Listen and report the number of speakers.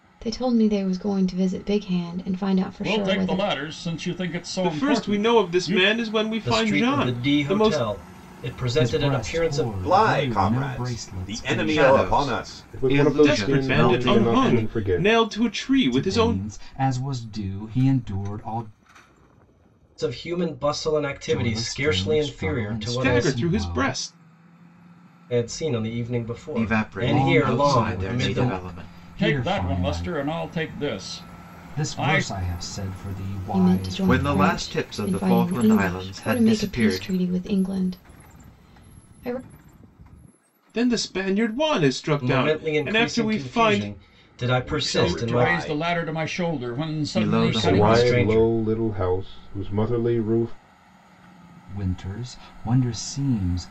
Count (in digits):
8